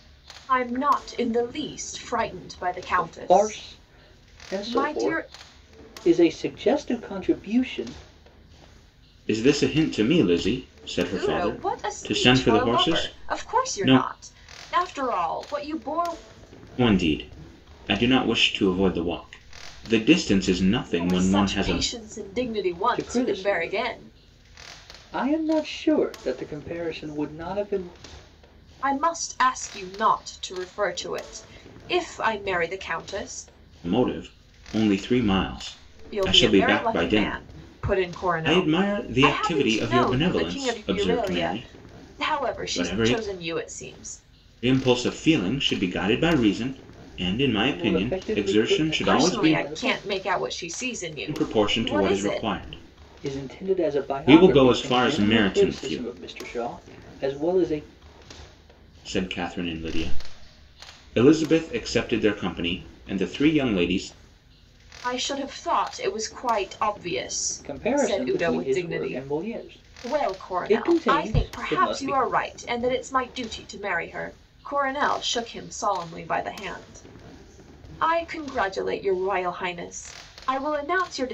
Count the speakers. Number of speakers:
3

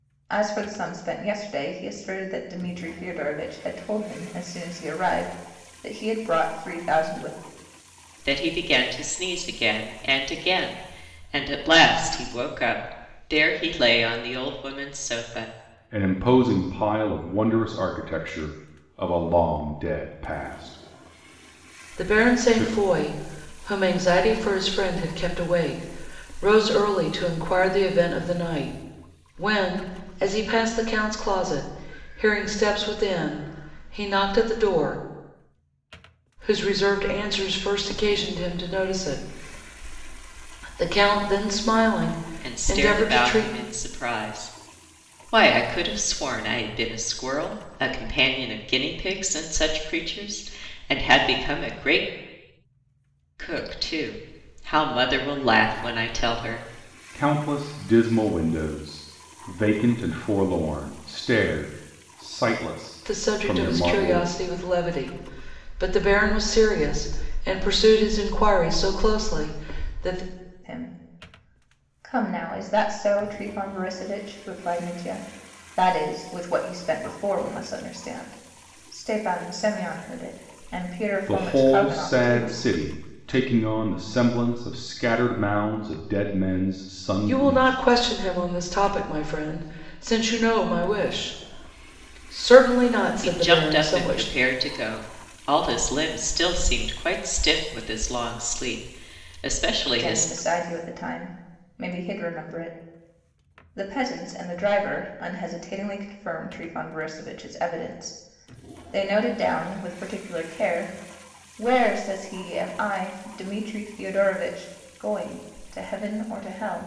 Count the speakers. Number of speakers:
4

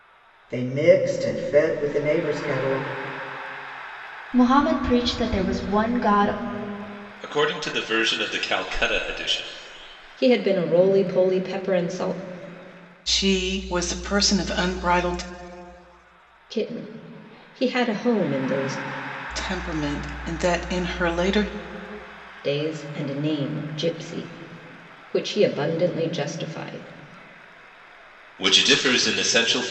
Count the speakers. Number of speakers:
5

